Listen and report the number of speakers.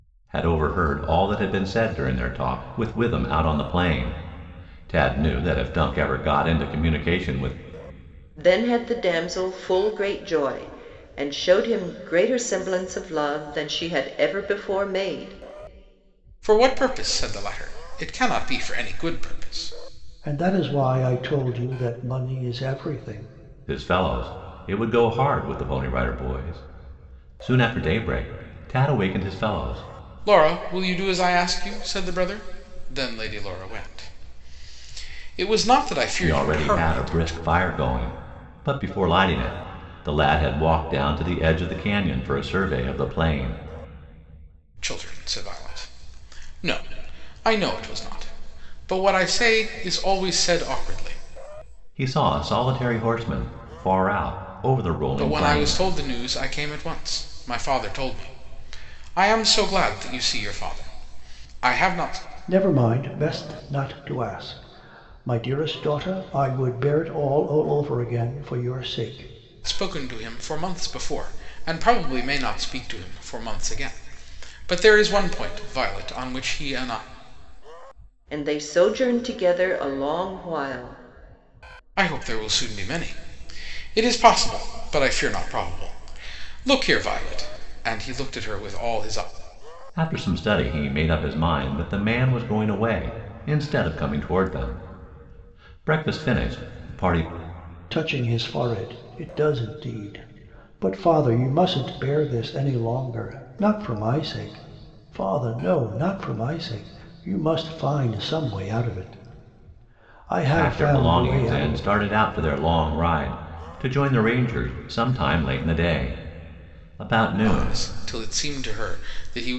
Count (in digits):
4